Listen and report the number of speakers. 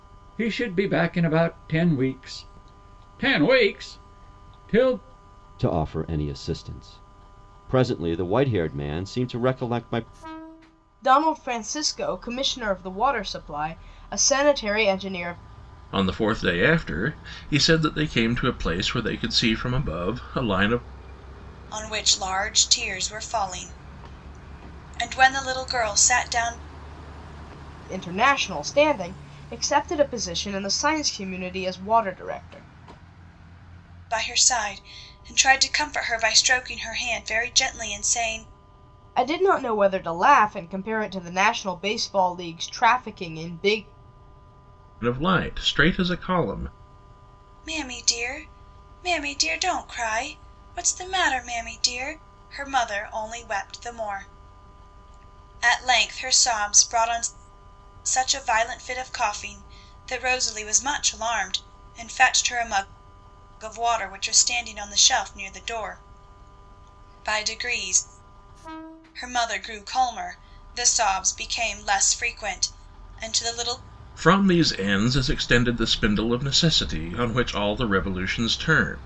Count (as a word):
five